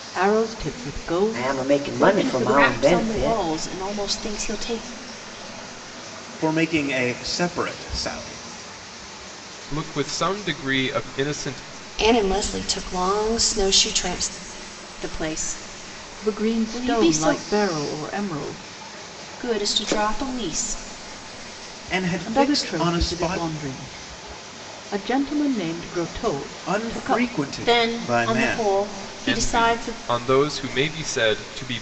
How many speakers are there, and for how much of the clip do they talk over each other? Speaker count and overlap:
6, about 23%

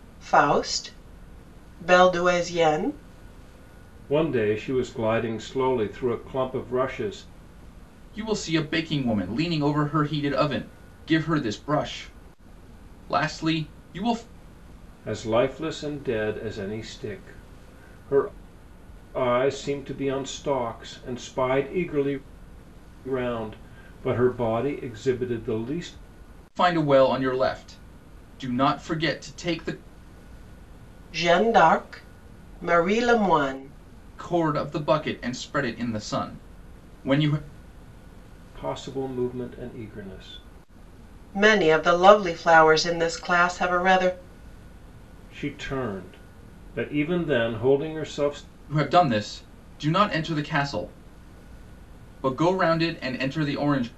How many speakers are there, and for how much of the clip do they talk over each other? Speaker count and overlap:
3, no overlap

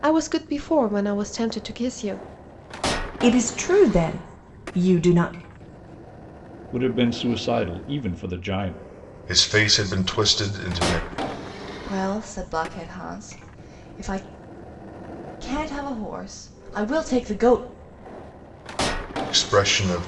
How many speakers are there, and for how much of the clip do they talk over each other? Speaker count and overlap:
5, no overlap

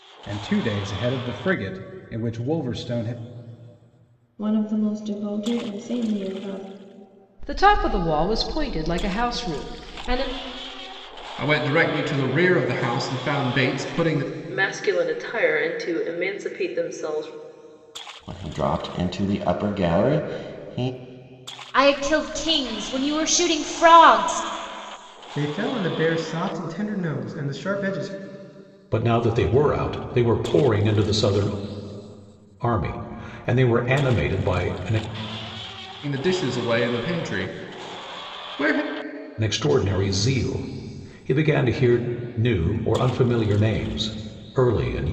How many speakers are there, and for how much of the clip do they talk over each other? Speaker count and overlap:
9, no overlap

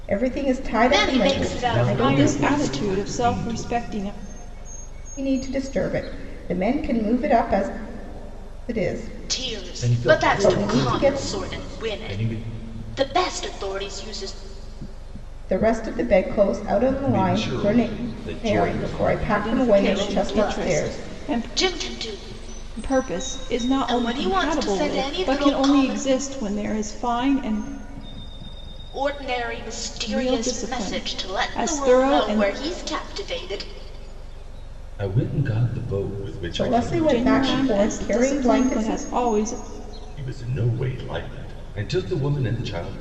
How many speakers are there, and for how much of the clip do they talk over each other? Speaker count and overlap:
4, about 40%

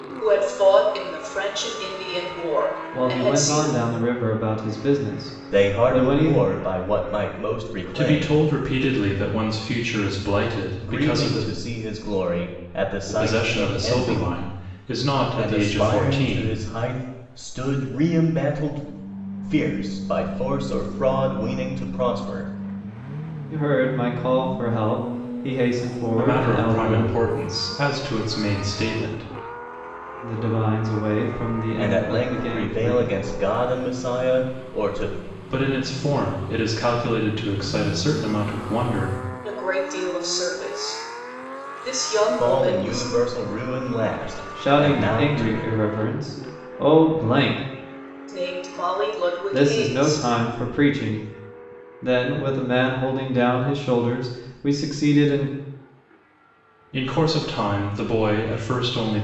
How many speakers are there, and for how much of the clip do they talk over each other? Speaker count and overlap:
4, about 18%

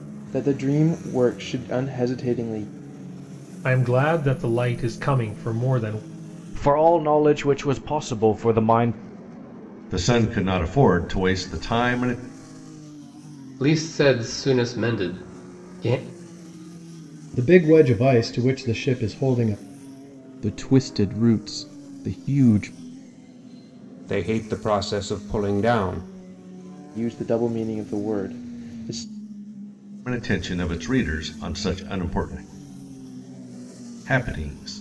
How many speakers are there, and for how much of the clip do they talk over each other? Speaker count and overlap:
8, no overlap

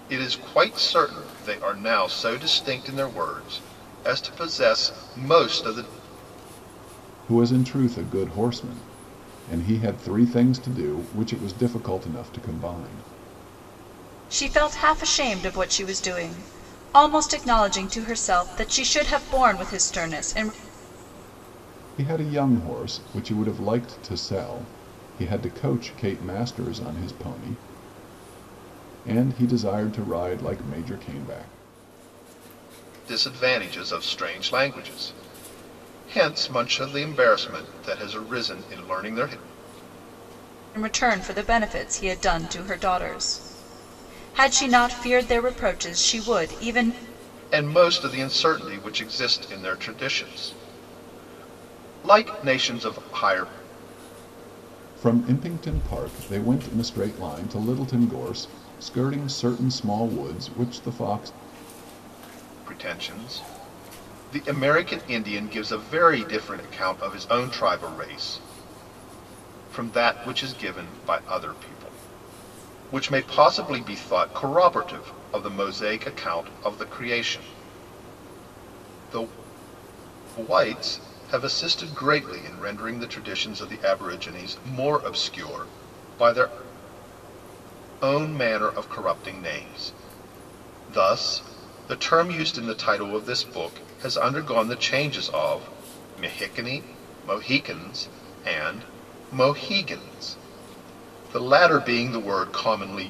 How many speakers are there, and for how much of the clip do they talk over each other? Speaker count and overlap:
3, no overlap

